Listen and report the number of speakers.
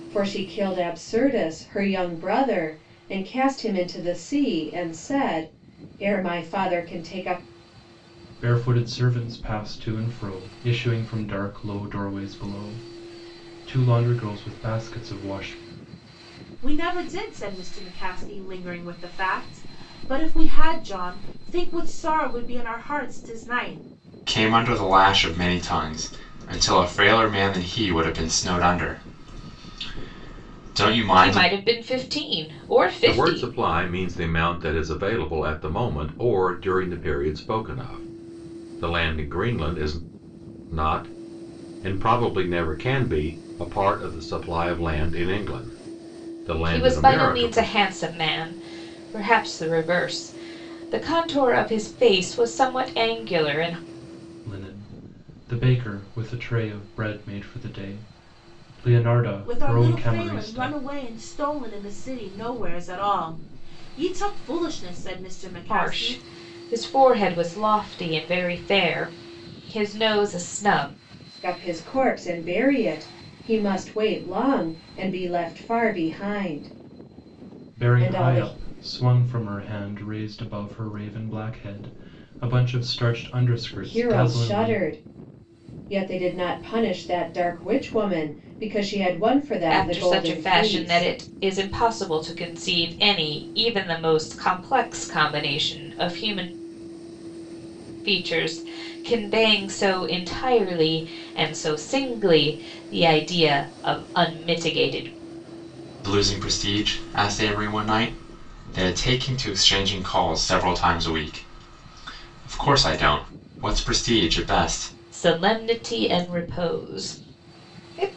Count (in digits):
6